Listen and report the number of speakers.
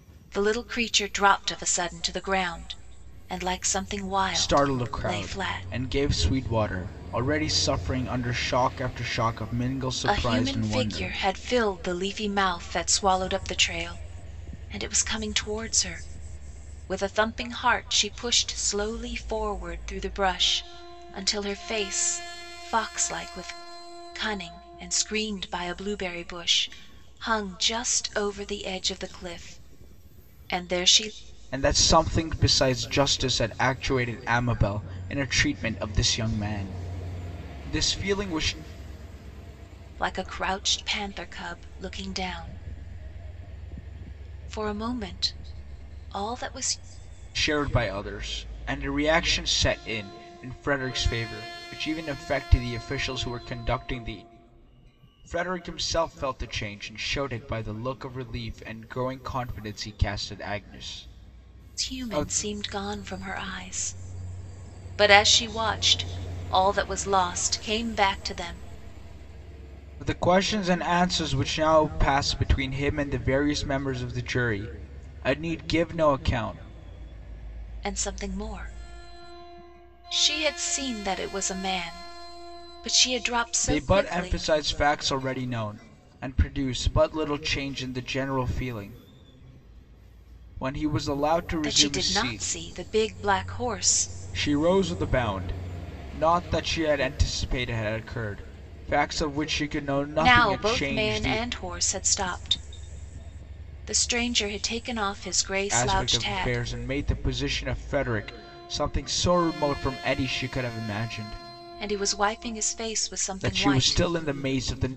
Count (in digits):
2